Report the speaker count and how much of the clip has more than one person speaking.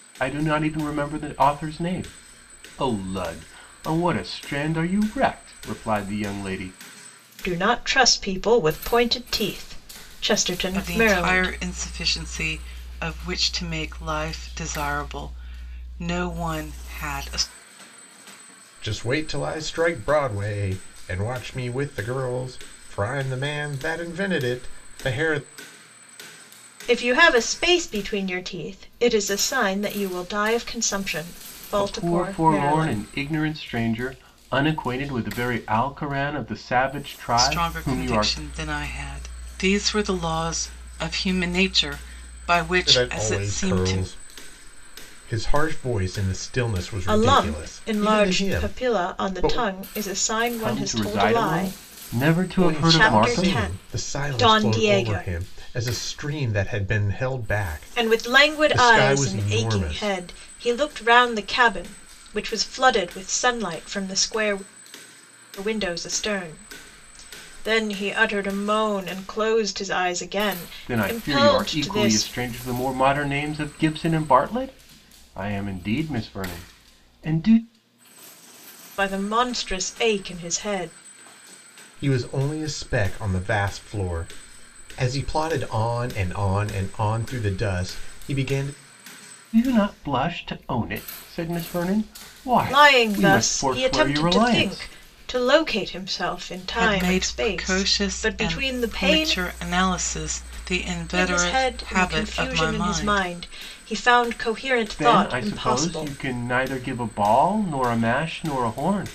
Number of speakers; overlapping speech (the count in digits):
4, about 21%